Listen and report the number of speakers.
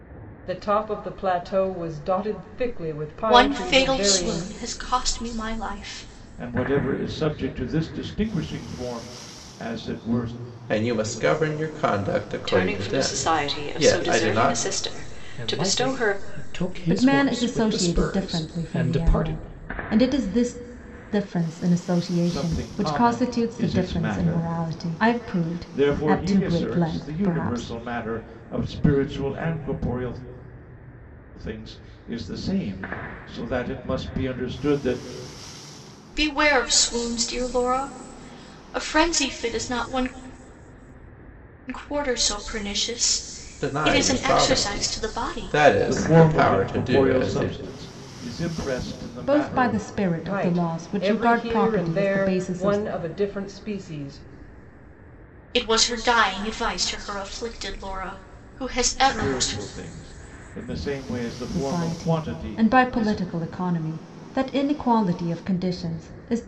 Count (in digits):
7